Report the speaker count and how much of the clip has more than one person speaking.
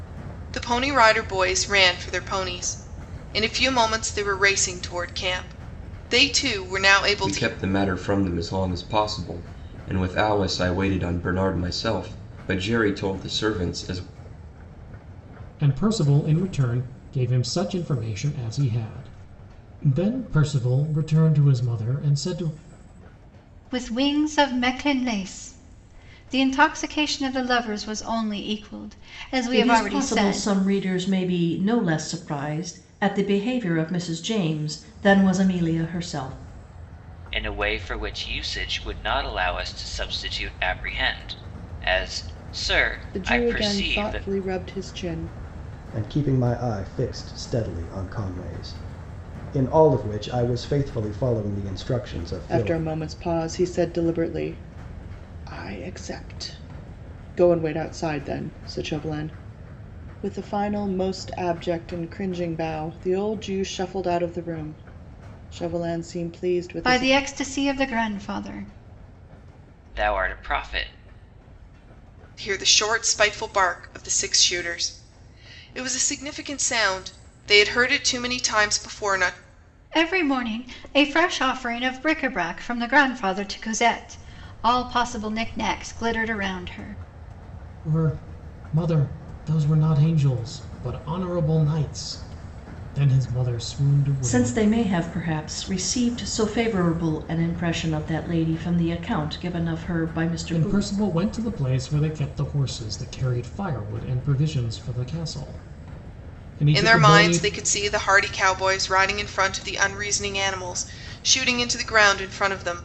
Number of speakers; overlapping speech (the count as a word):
eight, about 4%